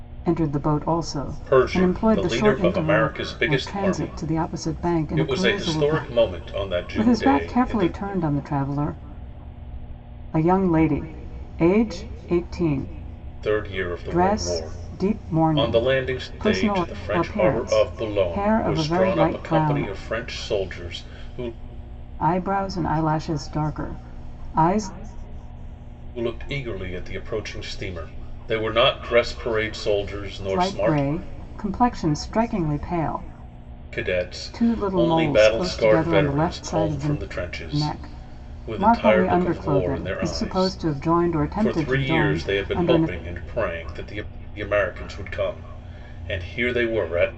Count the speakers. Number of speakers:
two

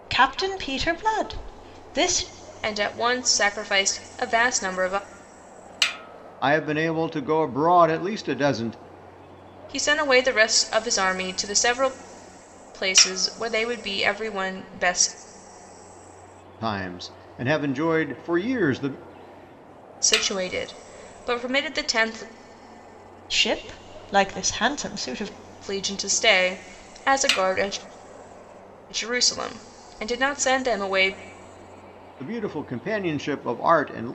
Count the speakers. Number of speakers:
three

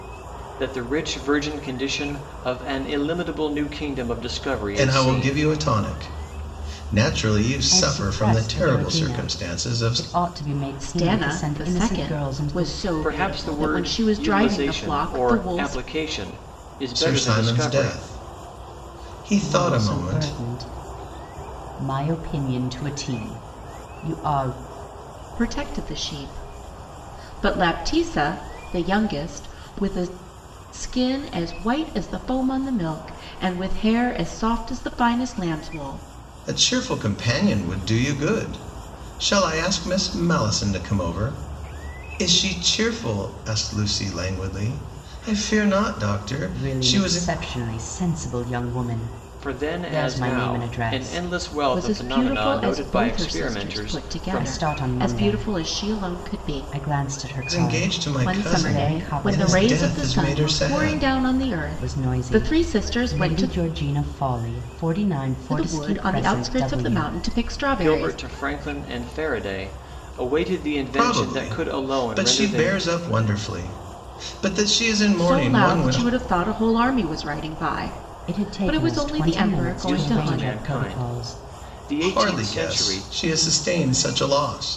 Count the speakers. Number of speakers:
four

